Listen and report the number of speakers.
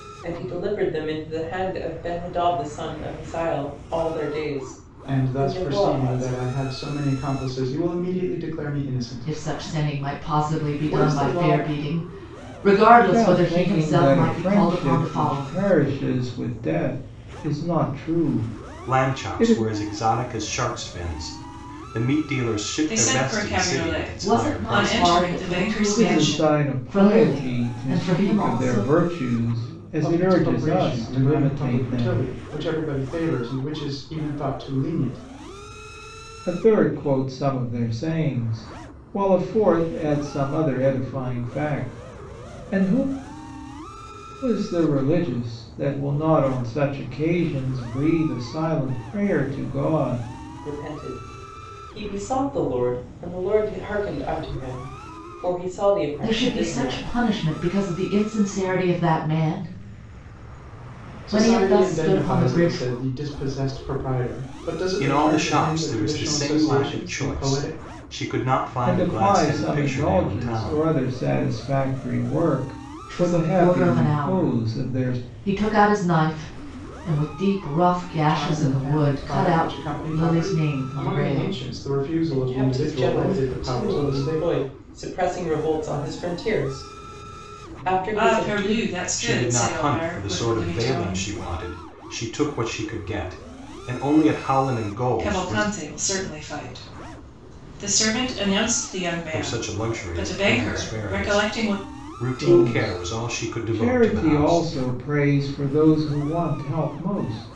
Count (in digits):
6